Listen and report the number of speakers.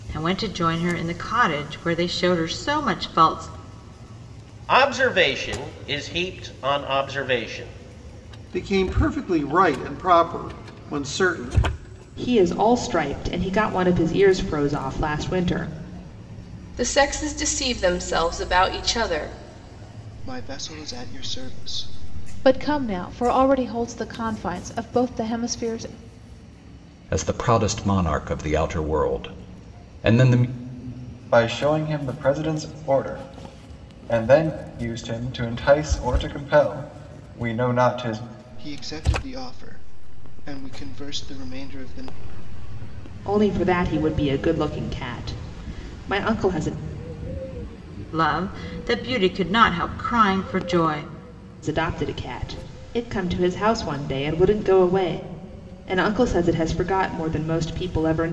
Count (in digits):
9